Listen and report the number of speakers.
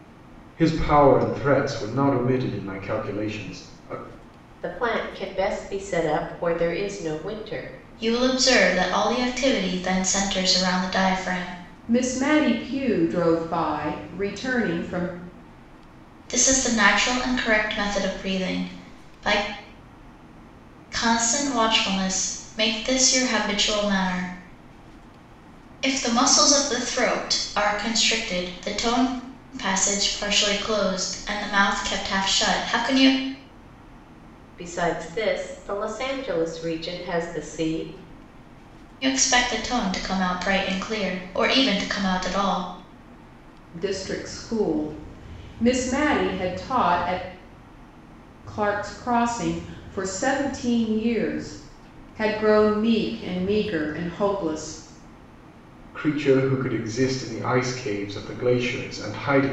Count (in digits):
4